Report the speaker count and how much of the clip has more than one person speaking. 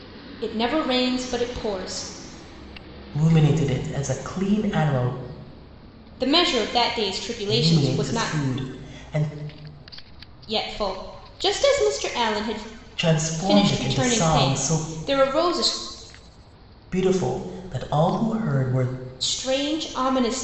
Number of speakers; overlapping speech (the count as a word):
two, about 12%